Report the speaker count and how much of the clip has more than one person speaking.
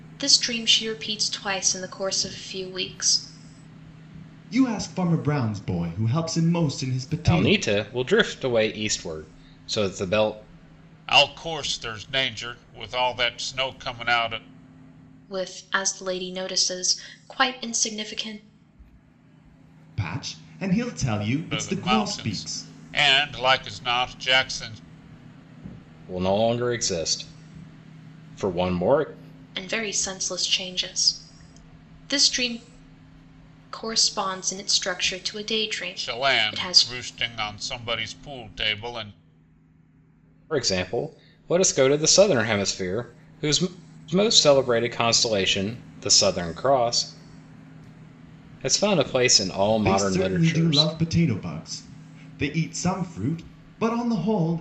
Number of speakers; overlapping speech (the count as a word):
four, about 7%